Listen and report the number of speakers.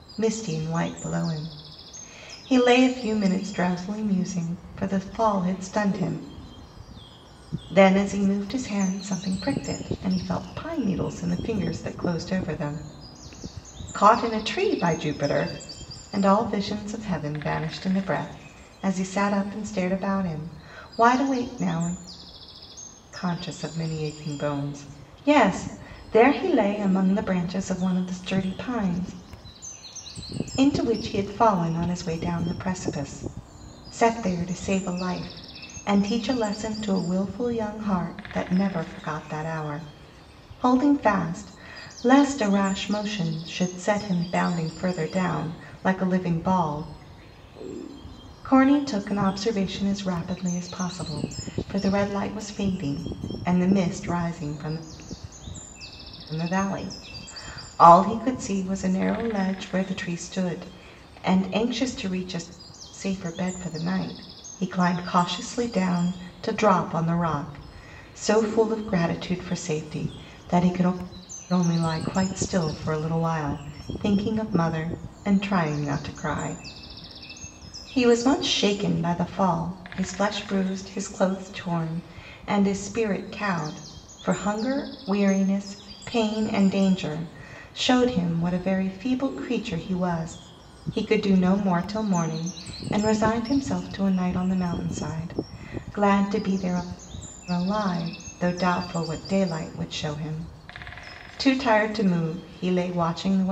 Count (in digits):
1